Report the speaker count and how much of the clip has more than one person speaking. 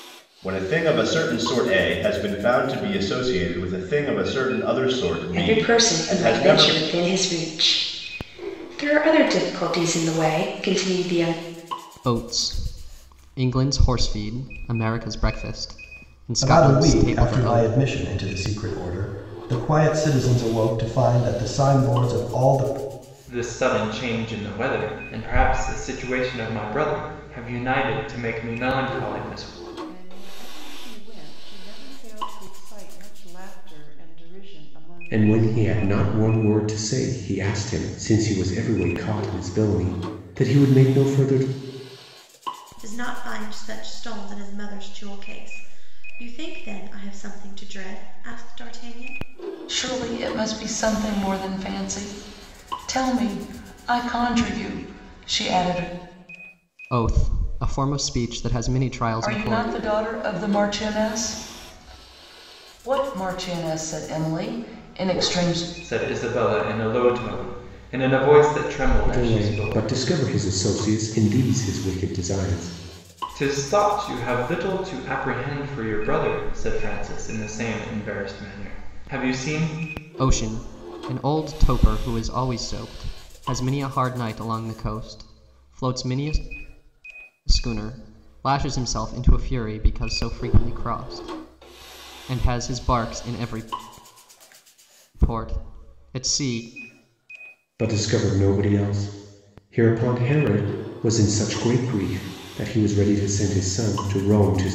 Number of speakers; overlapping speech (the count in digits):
9, about 6%